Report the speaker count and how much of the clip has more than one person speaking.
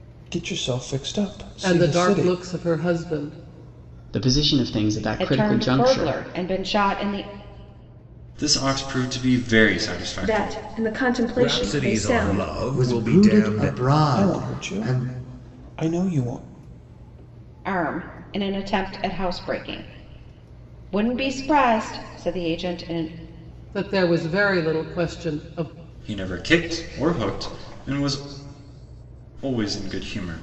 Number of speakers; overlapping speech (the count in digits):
8, about 18%